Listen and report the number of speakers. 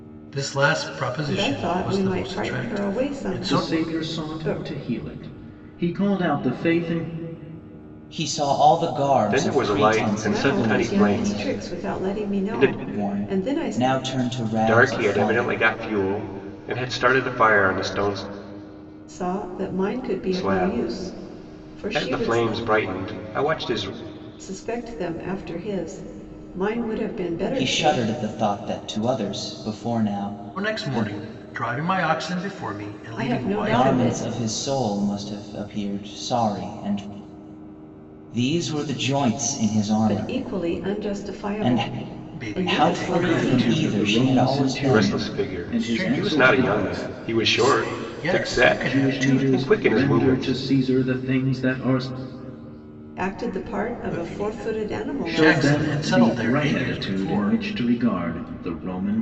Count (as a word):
five